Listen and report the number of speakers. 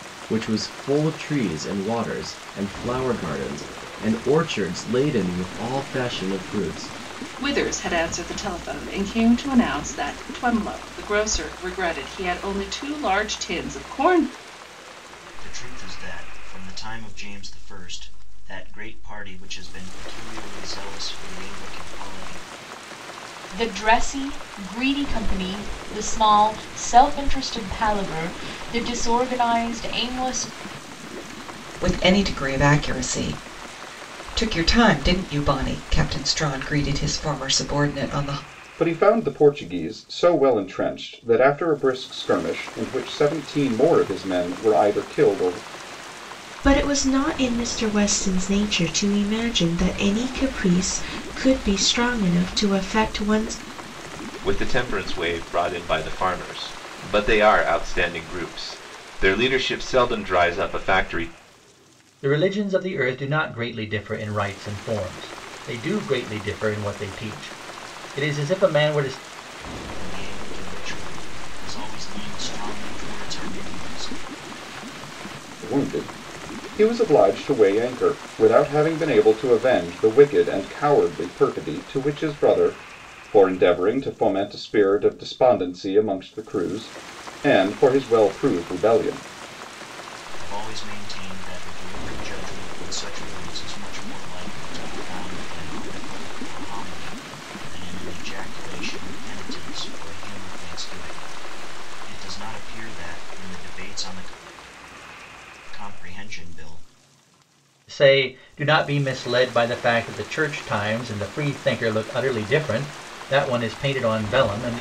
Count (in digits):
9